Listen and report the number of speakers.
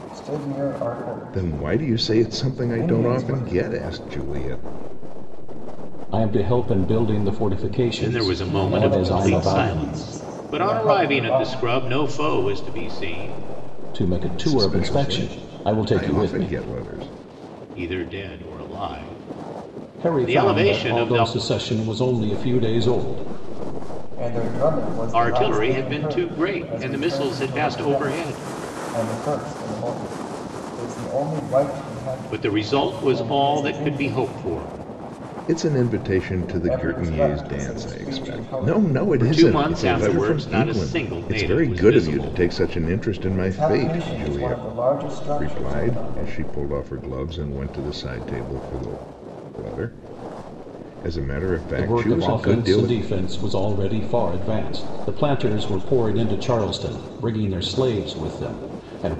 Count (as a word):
five